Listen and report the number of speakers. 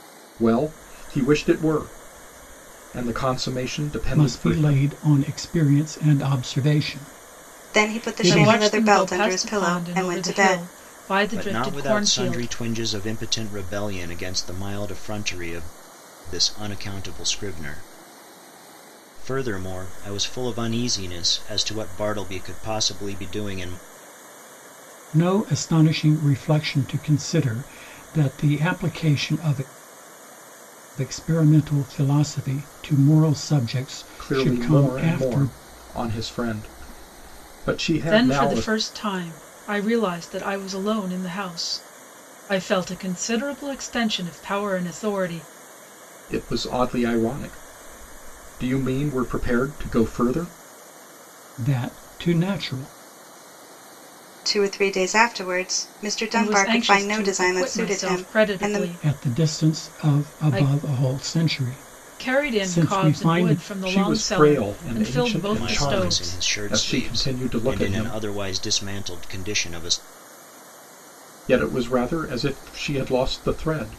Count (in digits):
5